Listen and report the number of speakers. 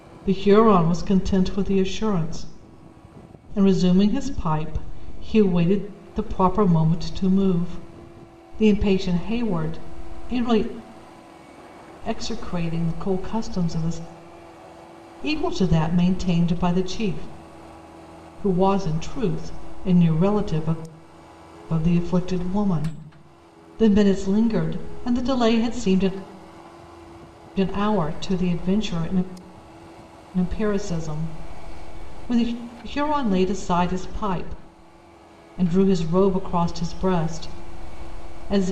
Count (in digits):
1